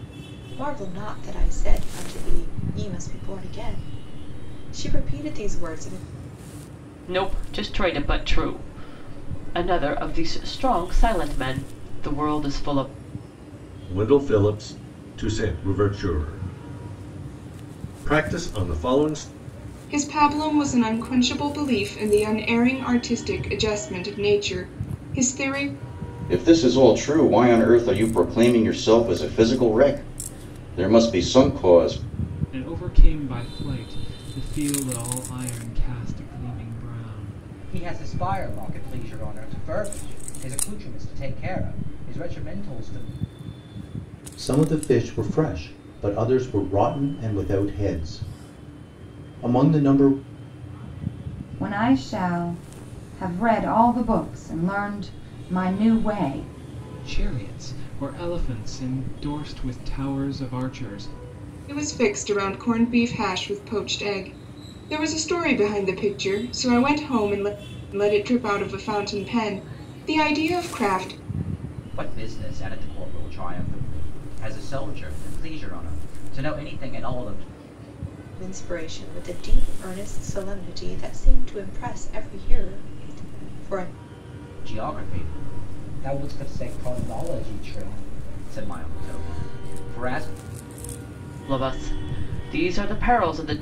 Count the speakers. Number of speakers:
nine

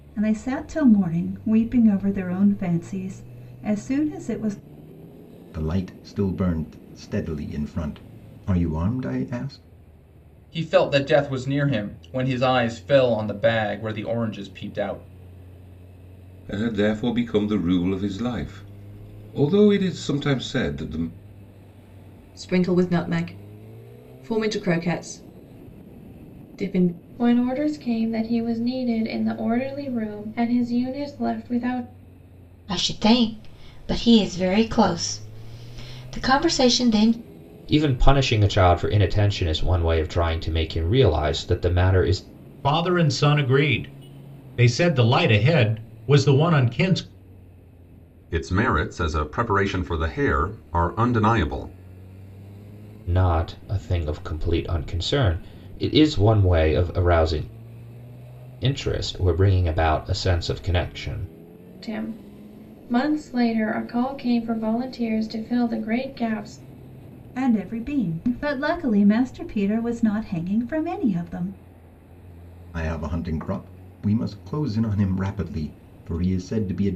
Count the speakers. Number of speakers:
ten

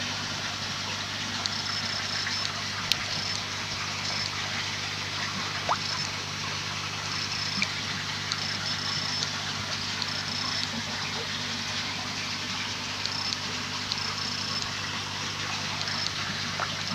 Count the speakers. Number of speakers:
zero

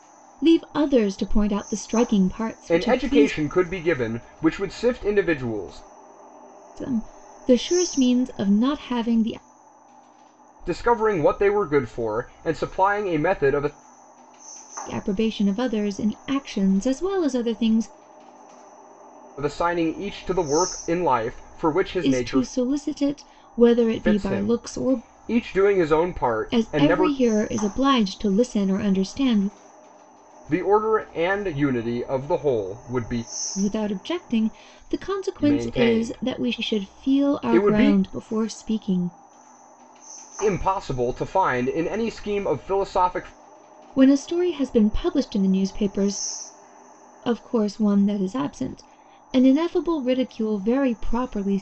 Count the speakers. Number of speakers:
two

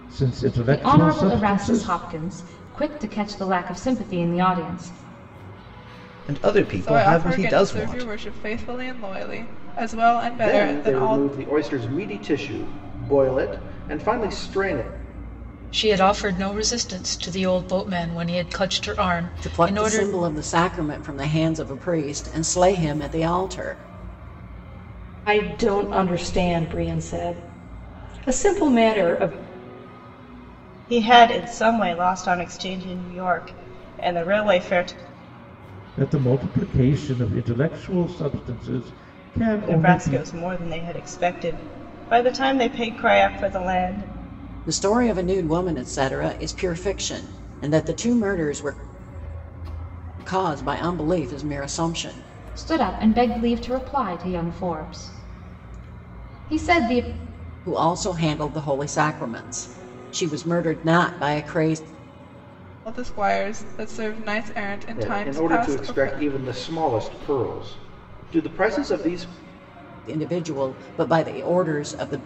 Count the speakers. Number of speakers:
nine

